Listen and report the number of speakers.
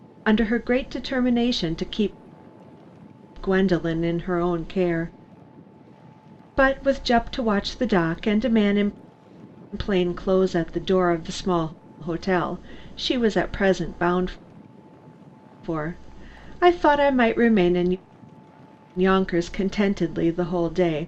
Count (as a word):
one